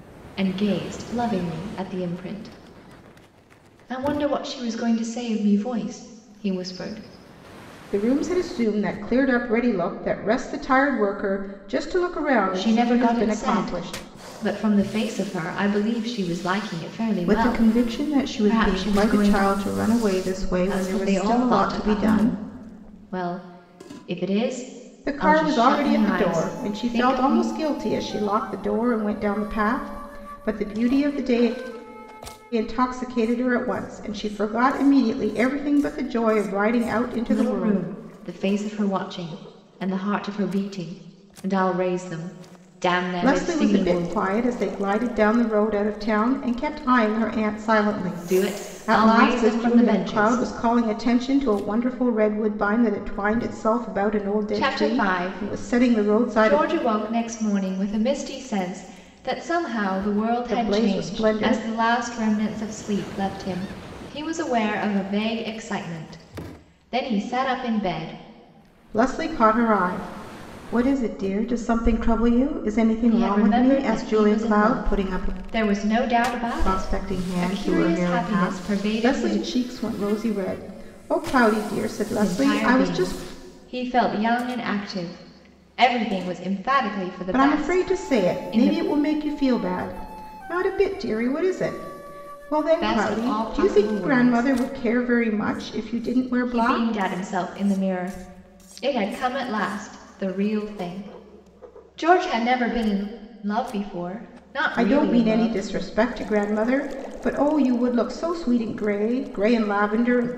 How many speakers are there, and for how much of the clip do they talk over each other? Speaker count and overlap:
two, about 24%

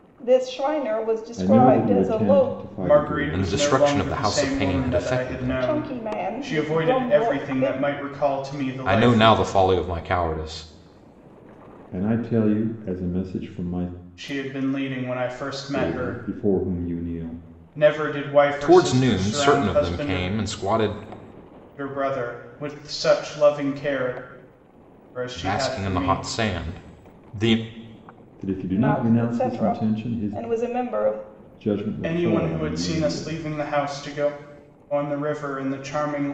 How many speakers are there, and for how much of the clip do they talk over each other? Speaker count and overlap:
four, about 37%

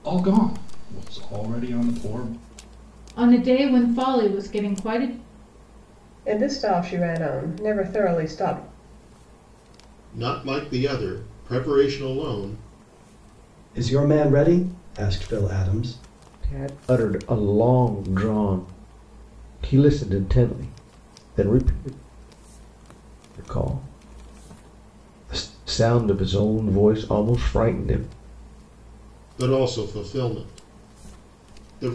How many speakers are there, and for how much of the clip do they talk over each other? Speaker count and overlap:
six, no overlap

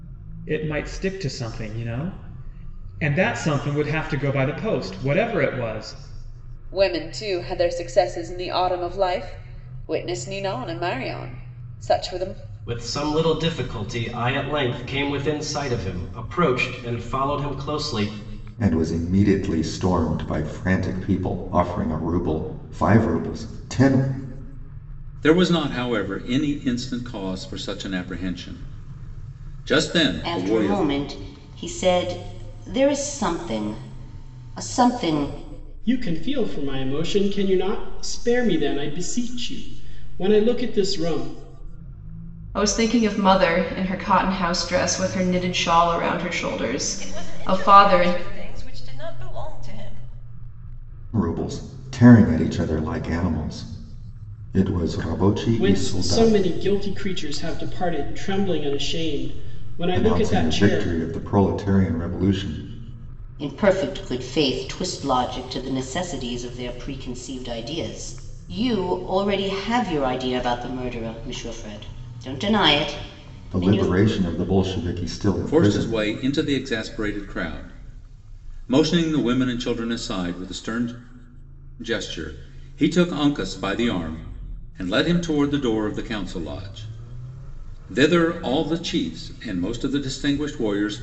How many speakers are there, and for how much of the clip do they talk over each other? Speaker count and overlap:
nine, about 5%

